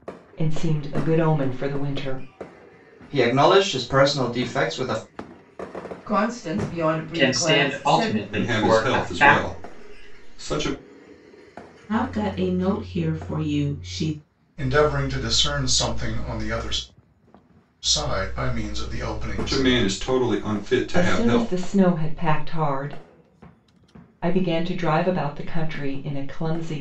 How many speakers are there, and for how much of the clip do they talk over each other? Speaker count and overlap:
7, about 13%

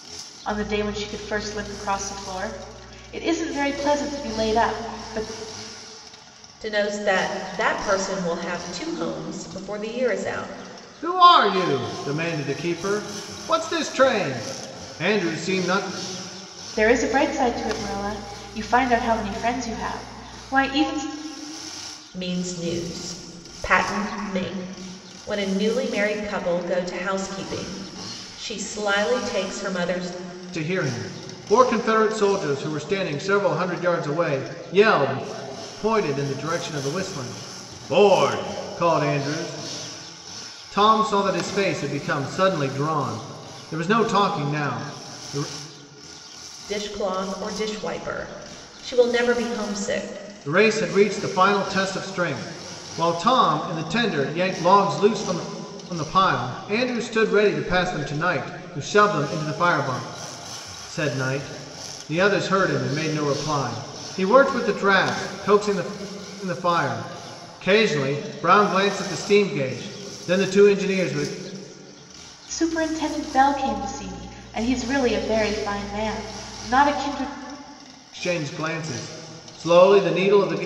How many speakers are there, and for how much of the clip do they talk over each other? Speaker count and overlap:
3, no overlap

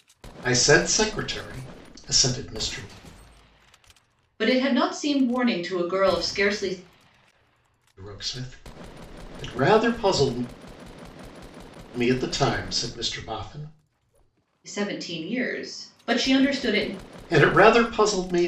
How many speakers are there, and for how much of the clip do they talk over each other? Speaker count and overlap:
2, no overlap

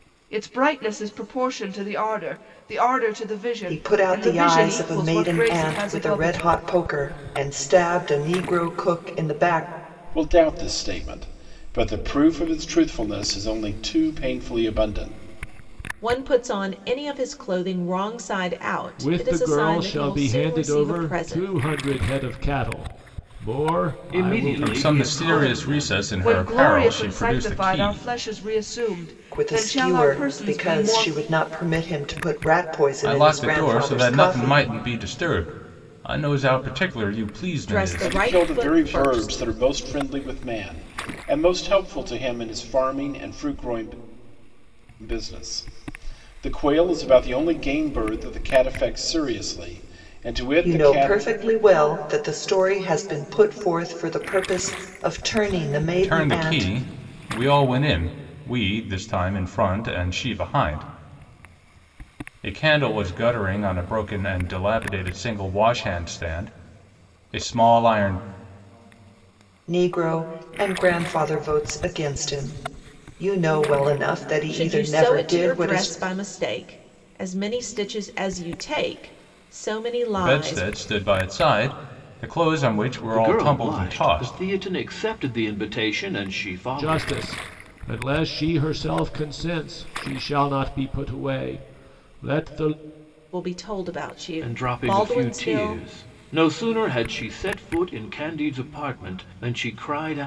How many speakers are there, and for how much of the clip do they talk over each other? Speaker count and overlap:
7, about 21%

